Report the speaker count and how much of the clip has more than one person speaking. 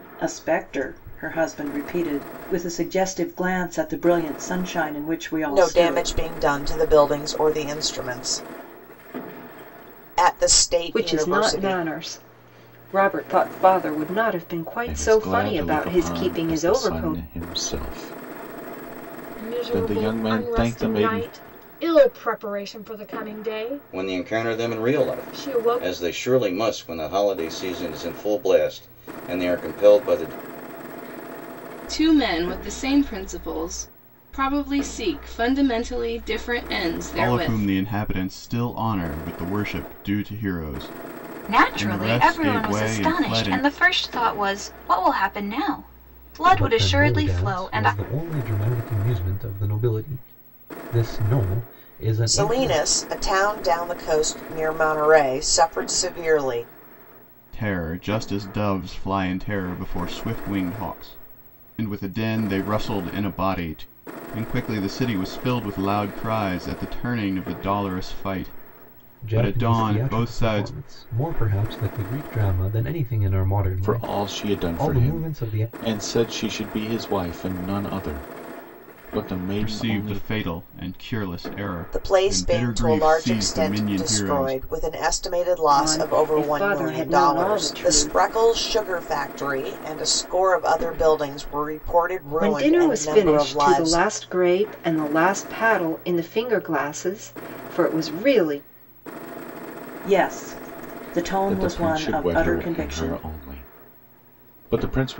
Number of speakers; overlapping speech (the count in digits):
10, about 25%